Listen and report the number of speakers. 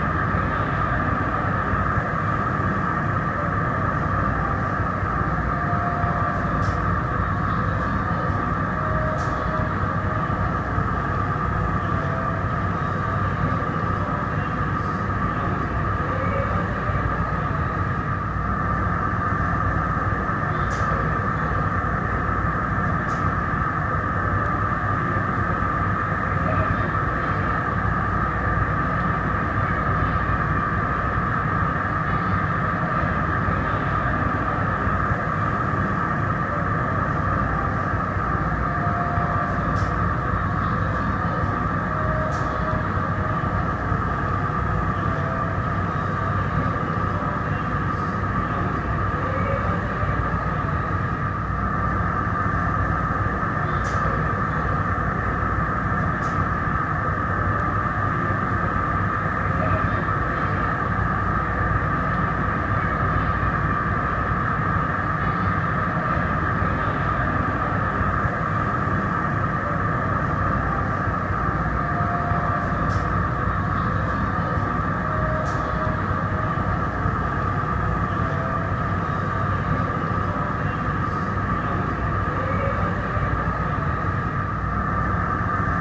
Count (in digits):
0